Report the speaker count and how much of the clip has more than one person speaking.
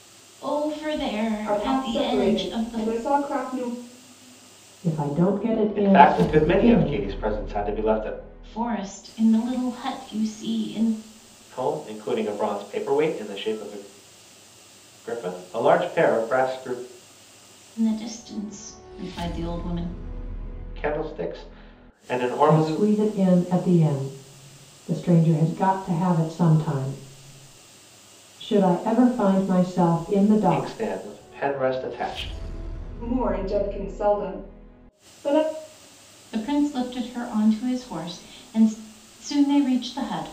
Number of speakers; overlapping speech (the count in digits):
4, about 9%